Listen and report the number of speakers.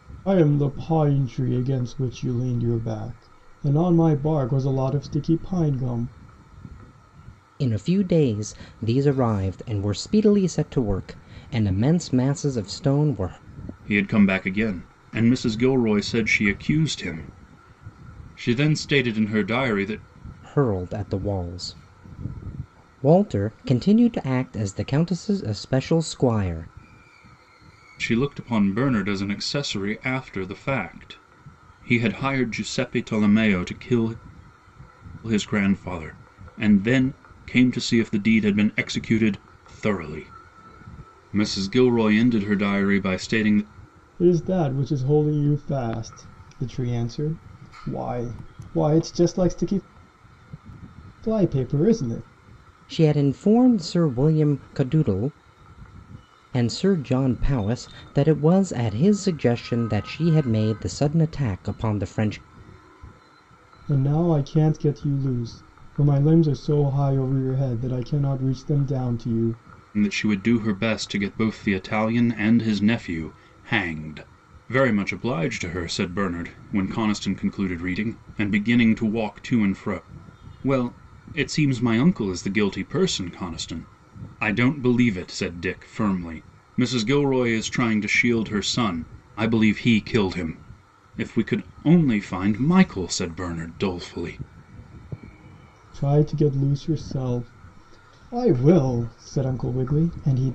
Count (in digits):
3